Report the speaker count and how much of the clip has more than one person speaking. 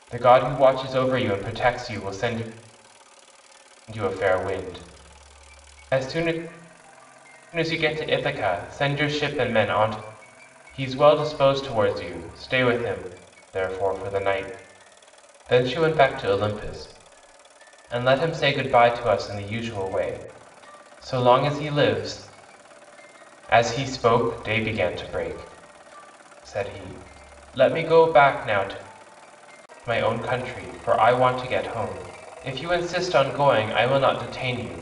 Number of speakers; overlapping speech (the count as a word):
one, no overlap